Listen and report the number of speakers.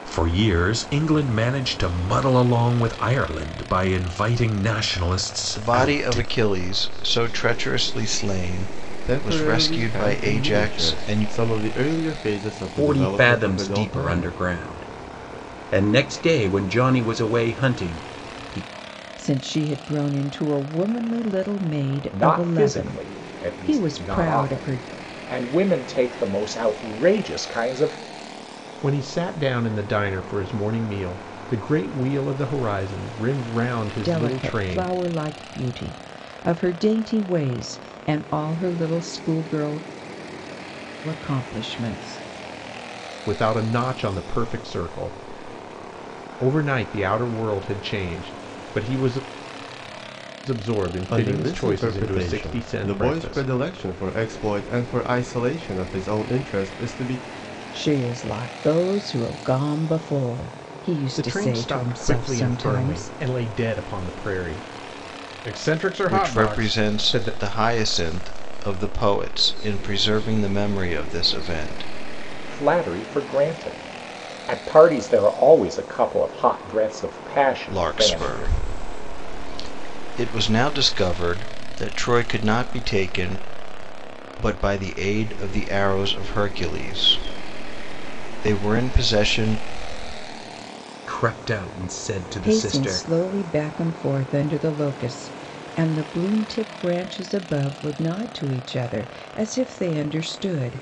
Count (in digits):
7